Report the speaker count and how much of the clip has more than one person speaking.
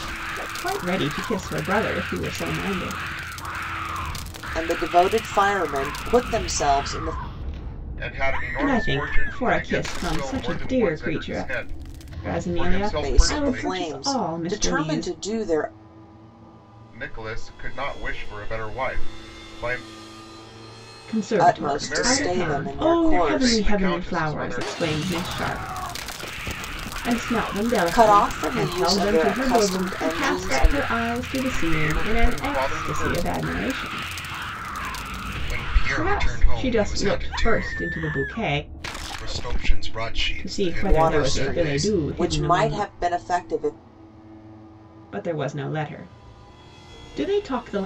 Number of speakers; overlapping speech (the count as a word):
three, about 40%